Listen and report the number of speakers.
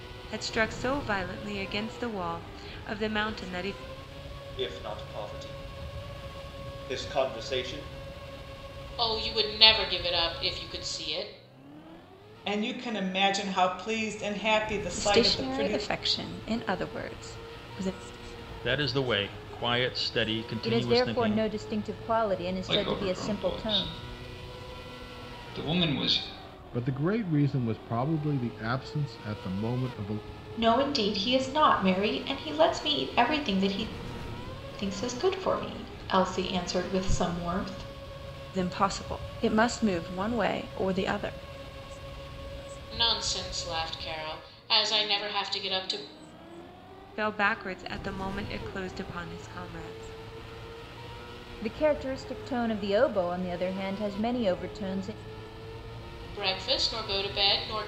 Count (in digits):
10